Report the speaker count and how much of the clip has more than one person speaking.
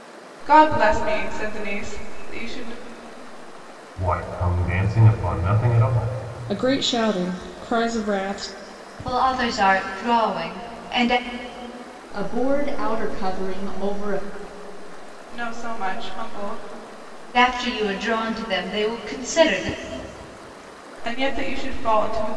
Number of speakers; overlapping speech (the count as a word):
five, no overlap